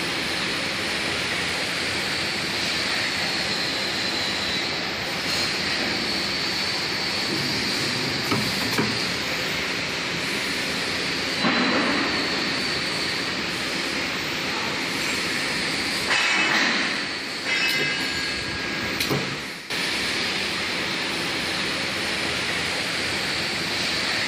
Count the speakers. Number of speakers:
zero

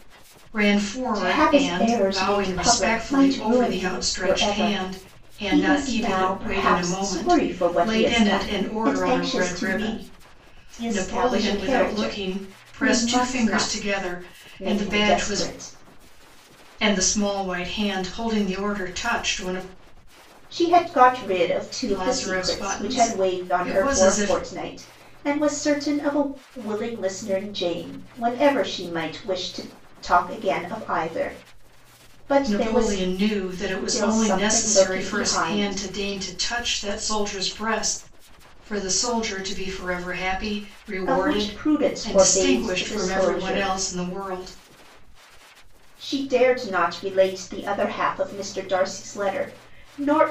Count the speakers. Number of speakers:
two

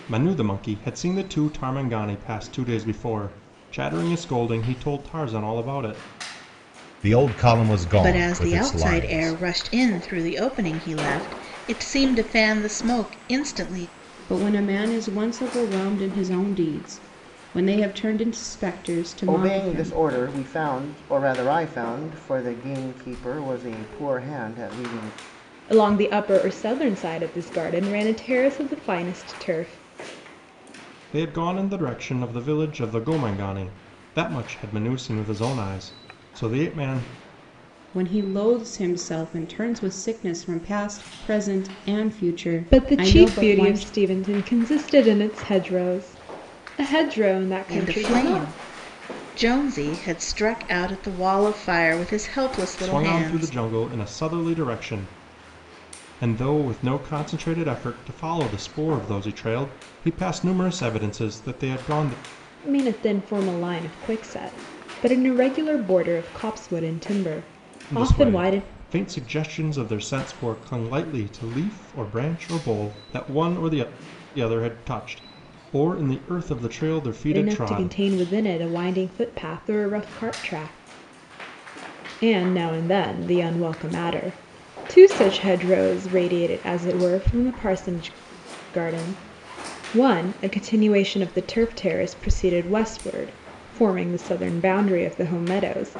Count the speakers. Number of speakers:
six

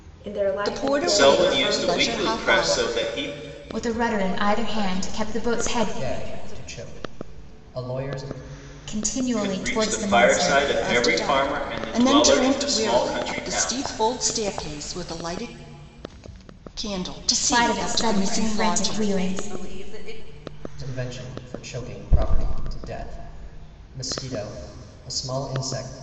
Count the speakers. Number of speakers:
six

